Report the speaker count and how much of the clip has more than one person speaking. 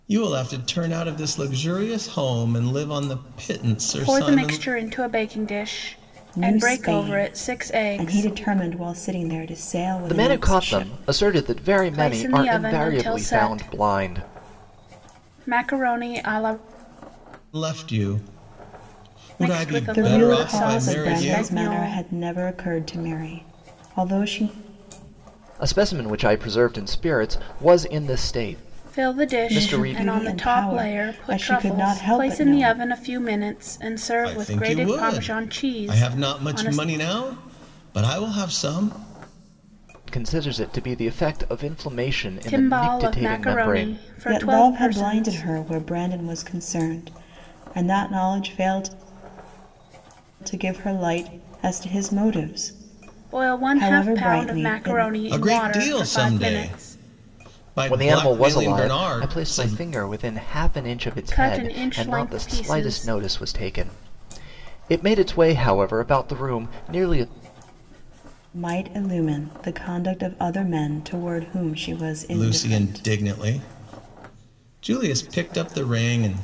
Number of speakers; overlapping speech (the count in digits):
4, about 34%